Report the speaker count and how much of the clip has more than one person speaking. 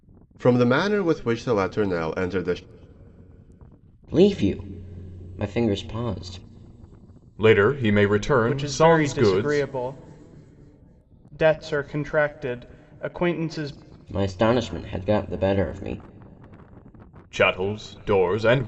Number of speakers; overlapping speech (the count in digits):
4, about 7%